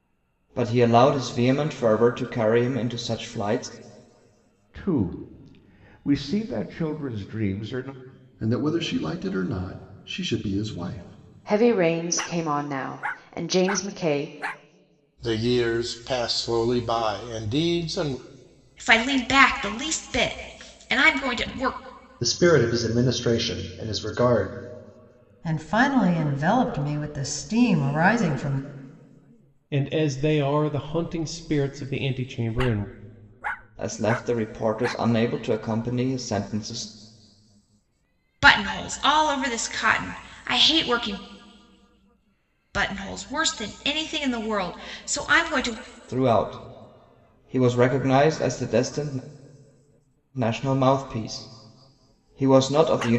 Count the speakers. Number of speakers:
nine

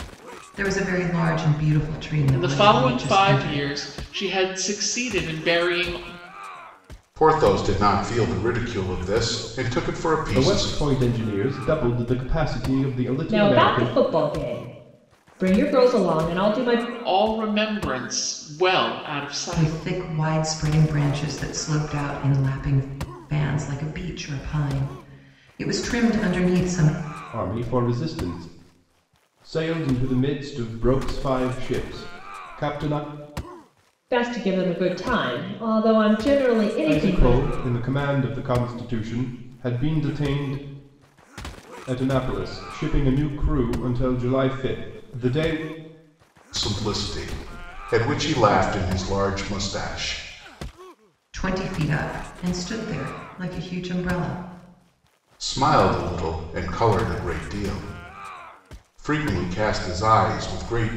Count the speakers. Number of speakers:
five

